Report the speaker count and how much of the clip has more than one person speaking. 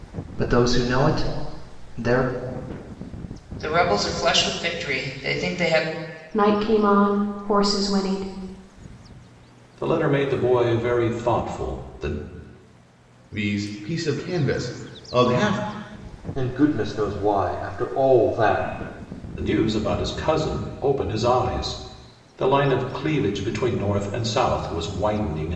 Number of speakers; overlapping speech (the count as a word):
six, no overlap